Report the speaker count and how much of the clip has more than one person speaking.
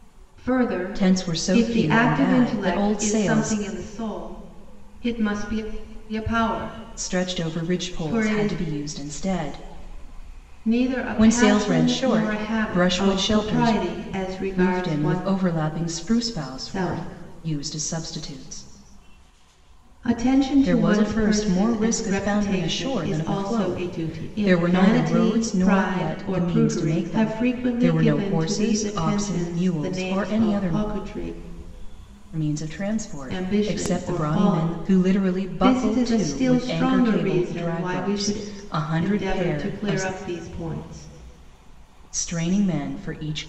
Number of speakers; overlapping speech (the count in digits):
2, about 57%